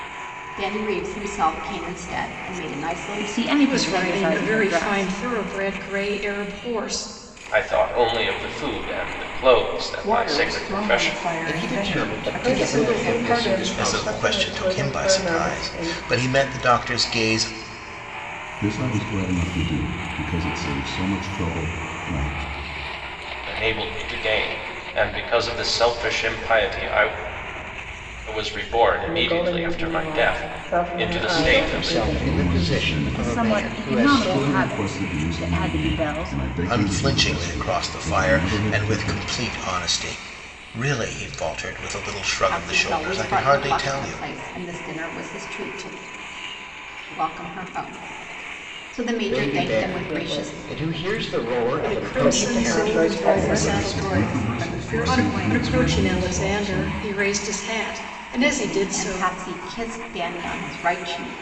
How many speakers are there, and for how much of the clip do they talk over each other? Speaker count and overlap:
9, about 46%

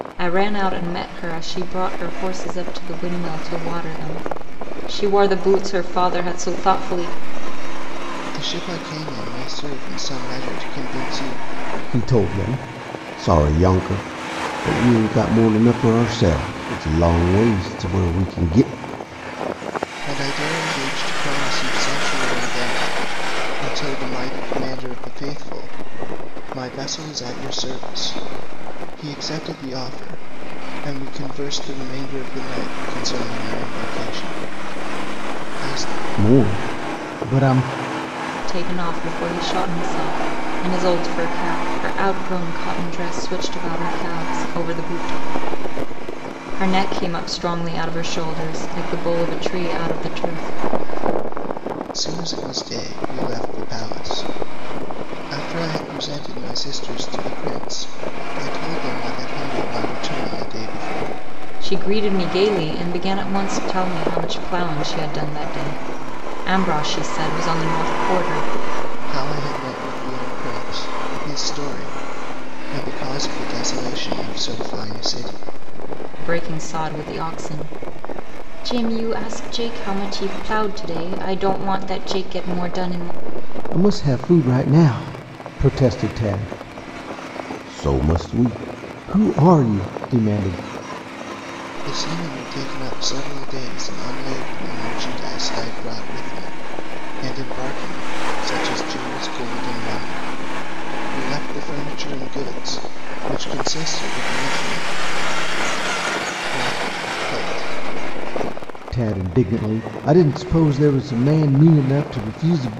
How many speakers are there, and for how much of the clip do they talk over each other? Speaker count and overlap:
3, no overlap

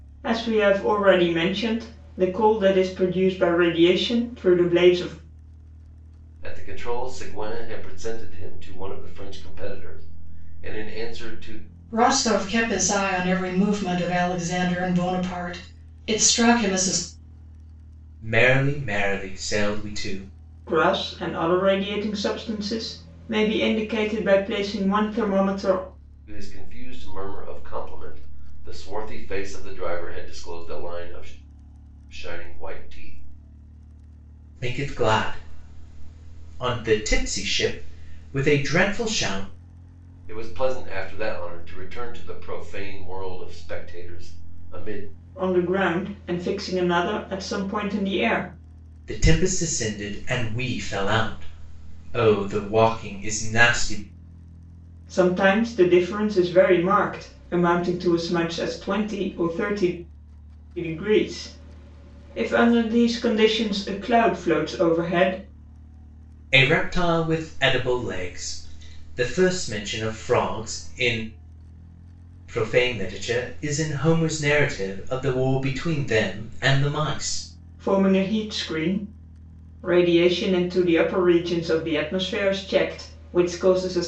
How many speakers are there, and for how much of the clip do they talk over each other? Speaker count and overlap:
4, no overlap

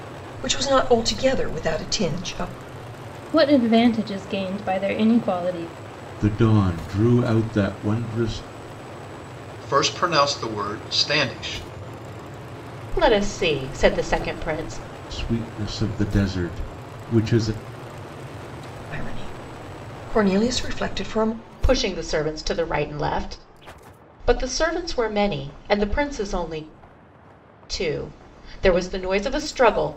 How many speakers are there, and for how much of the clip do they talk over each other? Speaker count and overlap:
5, no overlap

